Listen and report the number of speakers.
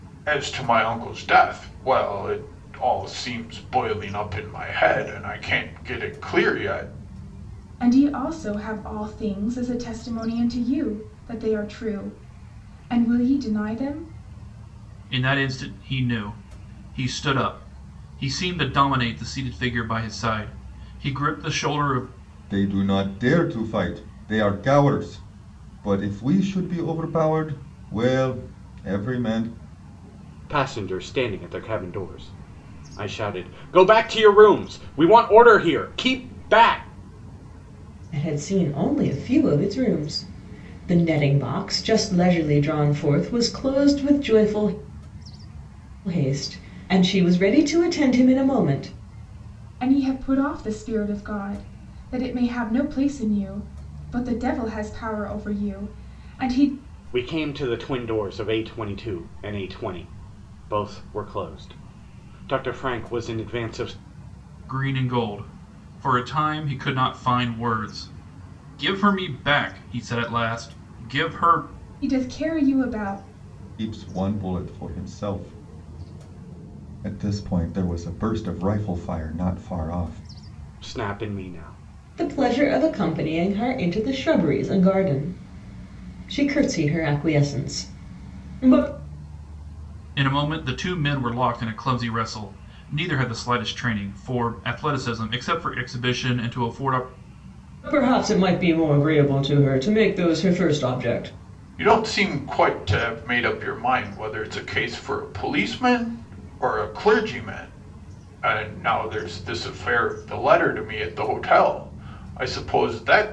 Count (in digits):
6